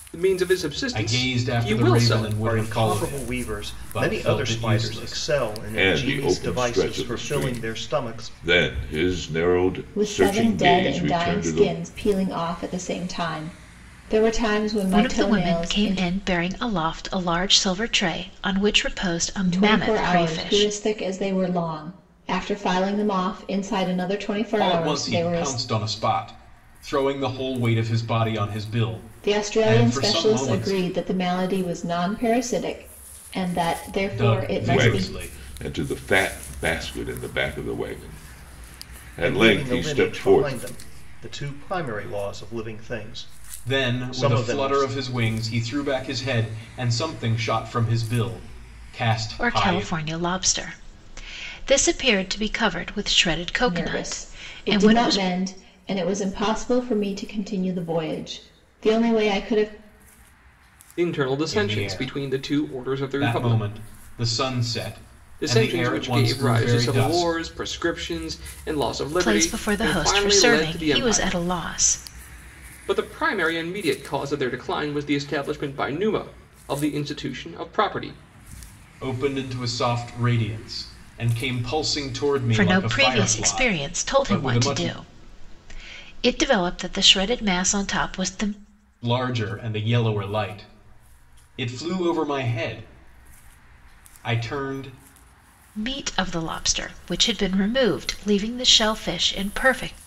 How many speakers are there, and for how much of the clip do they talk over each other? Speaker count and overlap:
six, about 29%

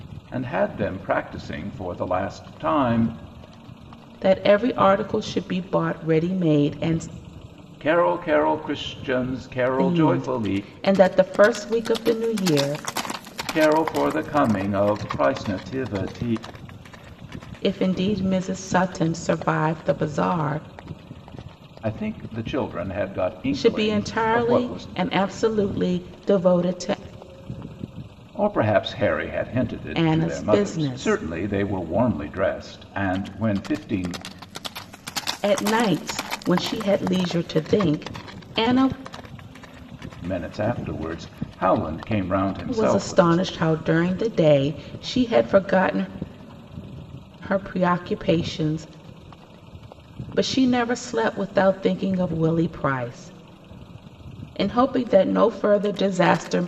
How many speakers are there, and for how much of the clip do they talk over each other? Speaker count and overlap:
two, about 8%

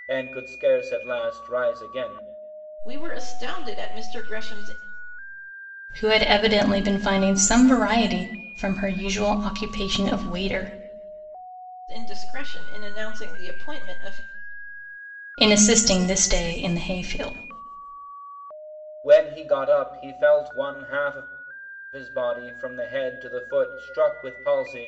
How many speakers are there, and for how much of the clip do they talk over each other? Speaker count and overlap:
three, no overlap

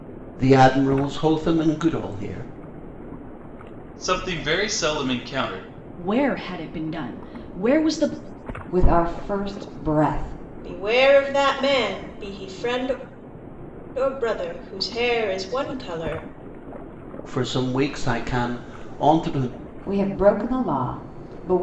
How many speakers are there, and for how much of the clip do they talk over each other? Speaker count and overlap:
five, no overlap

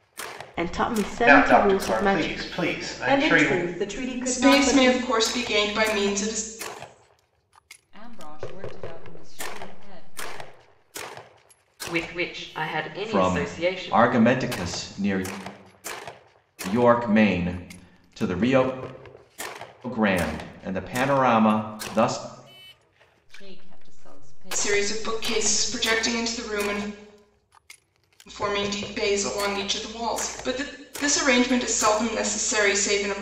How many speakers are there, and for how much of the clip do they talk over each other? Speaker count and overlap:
seven, about 14%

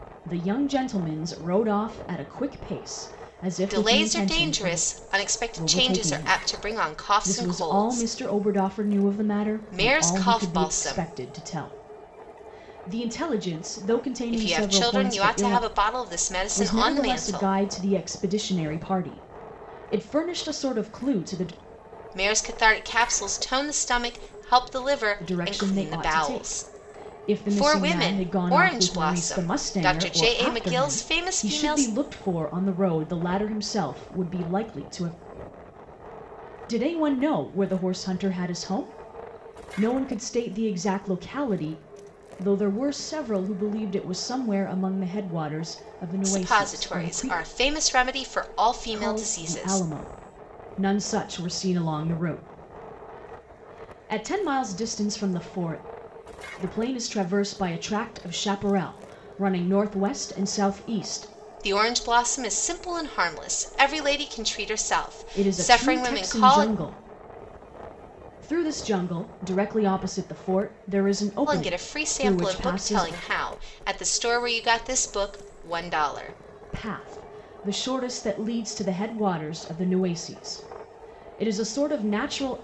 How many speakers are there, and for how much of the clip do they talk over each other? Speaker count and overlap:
two, about 23%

